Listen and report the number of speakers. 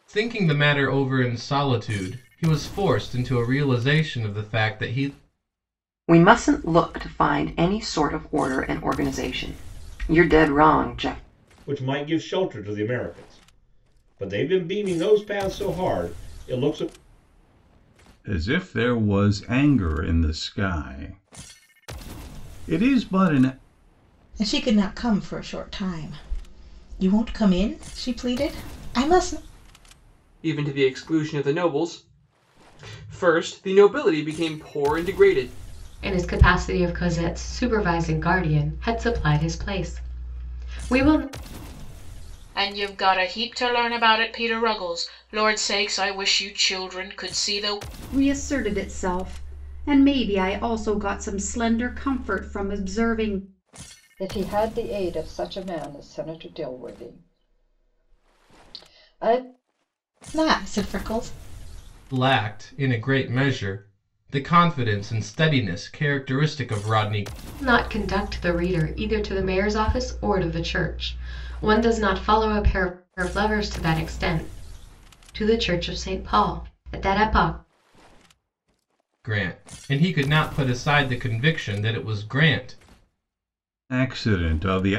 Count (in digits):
10